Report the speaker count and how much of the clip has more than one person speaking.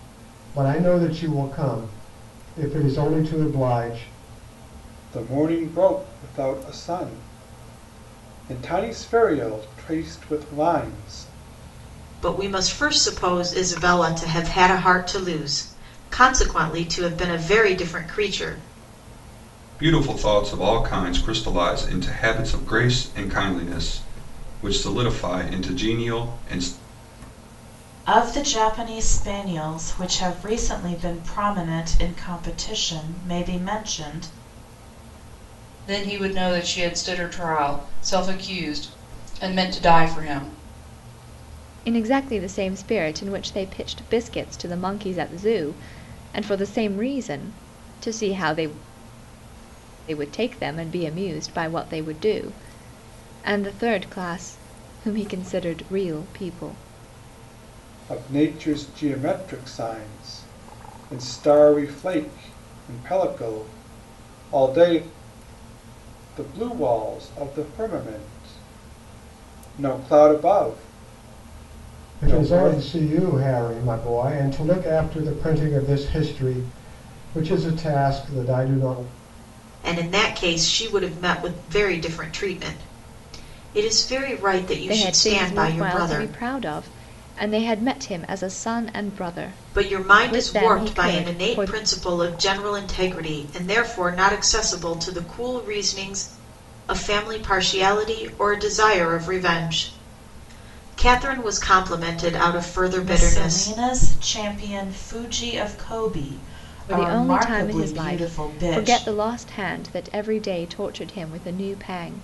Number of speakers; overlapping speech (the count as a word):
seven, about 6%